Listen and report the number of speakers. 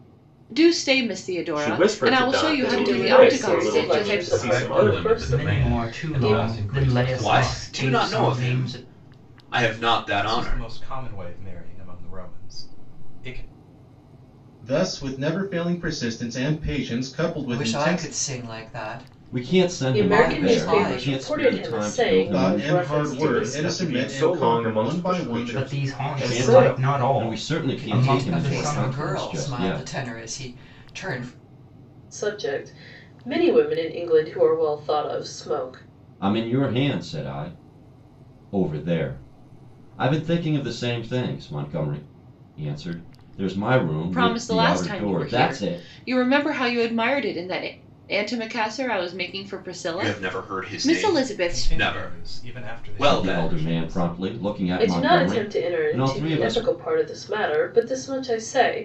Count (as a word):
ten